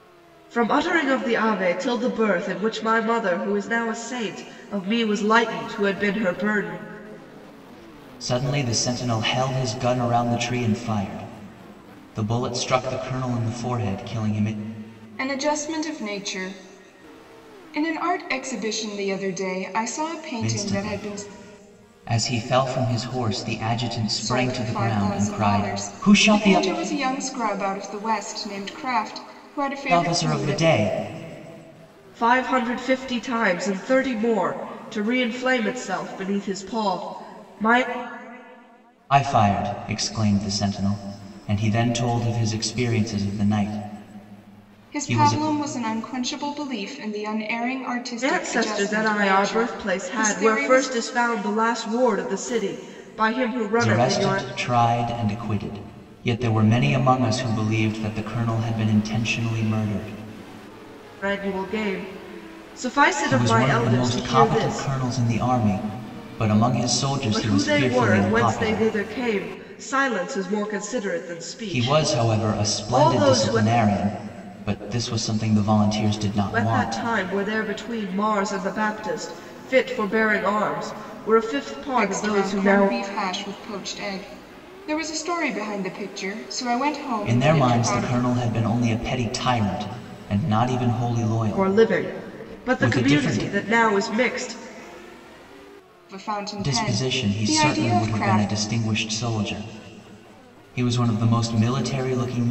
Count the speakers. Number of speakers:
3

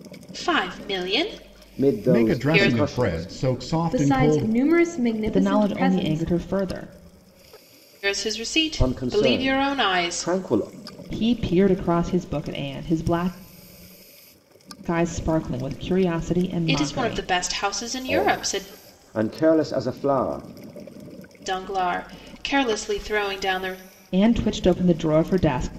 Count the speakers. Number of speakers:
5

